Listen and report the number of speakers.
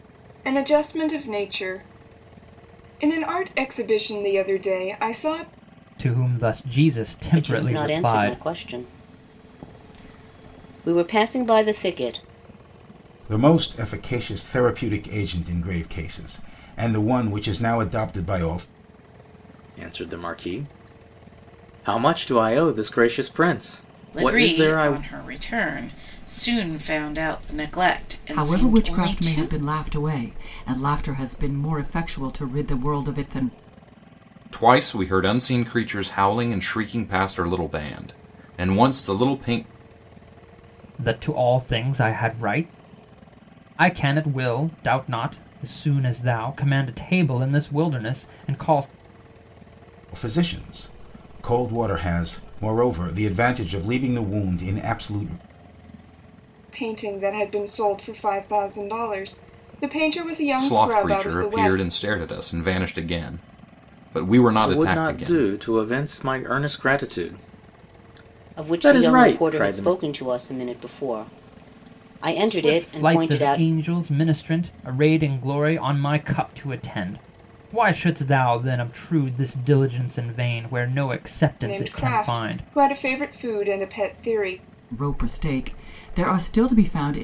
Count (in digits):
8